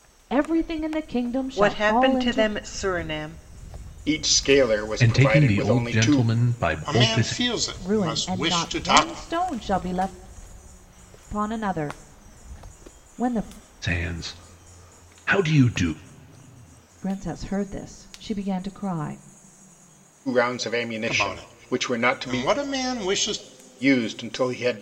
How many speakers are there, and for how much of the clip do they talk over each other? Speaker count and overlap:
five, about 23%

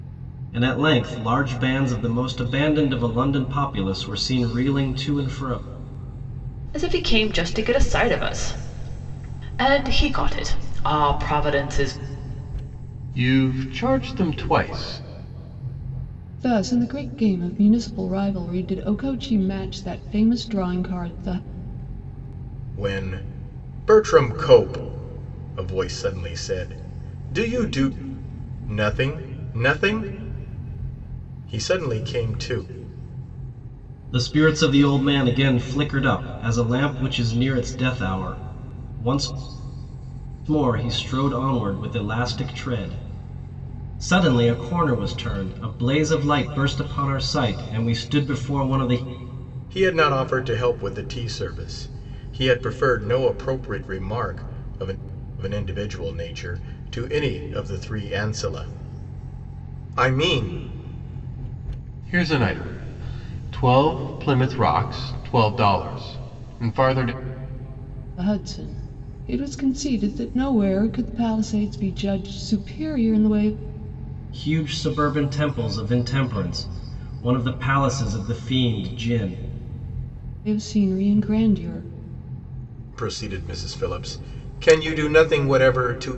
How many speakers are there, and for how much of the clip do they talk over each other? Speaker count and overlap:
five, no overlap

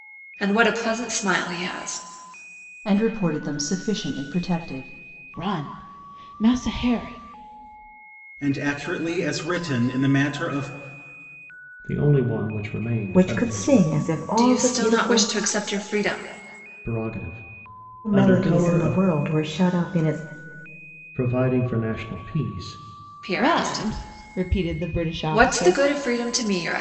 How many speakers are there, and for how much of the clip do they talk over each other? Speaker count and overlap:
six, about 14%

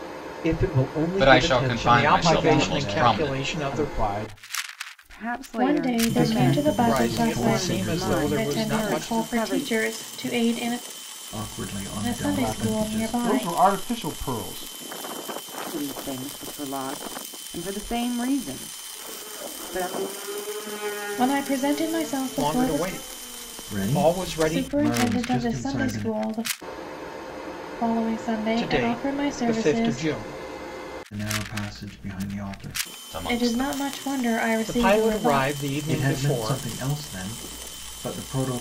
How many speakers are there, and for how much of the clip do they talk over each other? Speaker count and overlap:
seven, about 39%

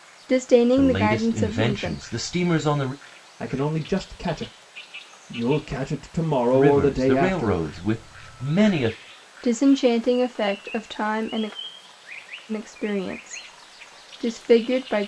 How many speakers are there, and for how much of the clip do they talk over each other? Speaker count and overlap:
three, about 16%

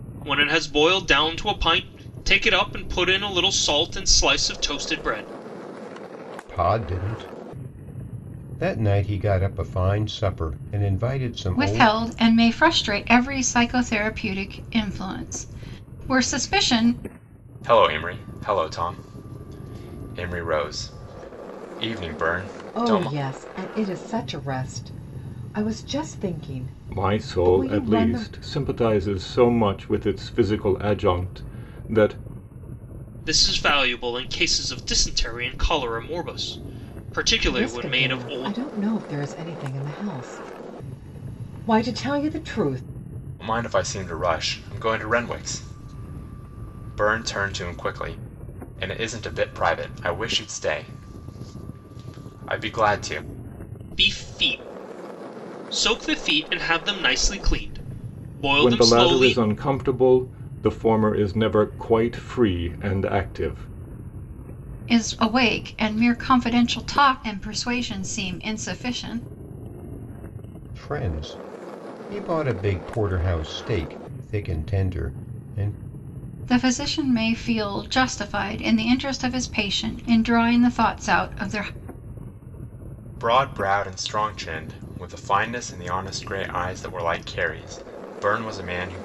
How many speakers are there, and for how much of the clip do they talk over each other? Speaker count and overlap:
six, about 5%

